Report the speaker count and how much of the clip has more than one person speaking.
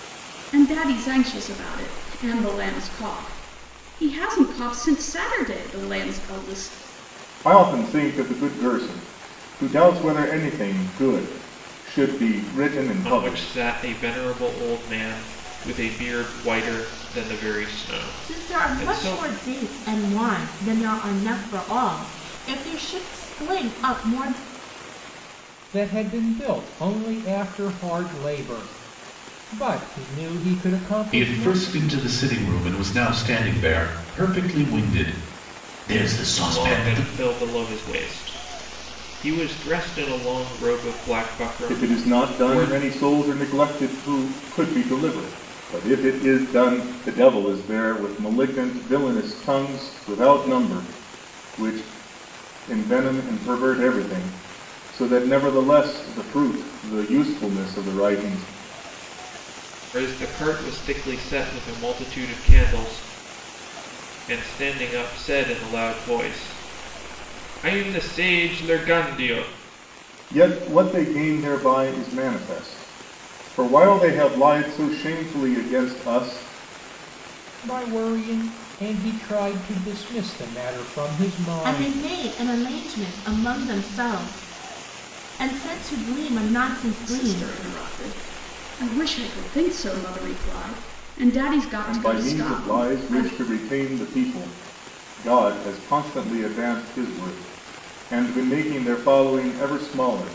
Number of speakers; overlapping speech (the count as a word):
six, about 7%